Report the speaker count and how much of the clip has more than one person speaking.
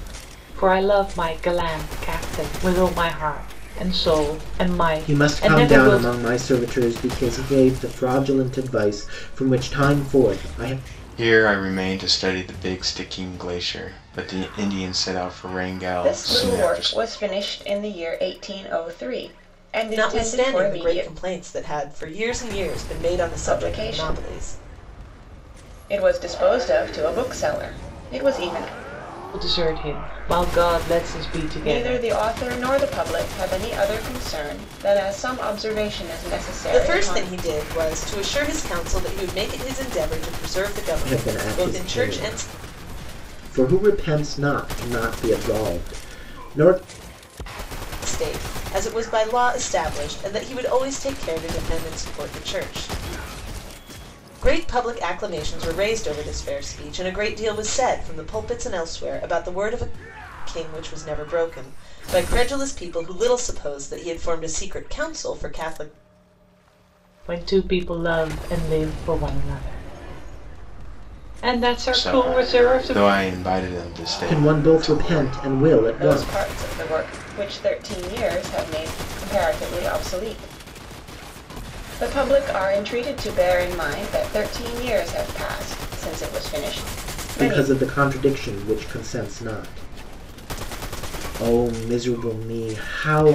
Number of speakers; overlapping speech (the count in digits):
5, about 11%